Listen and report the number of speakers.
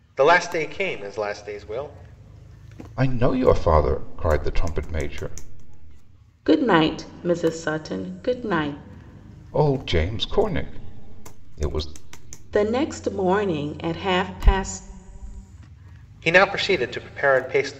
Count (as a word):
three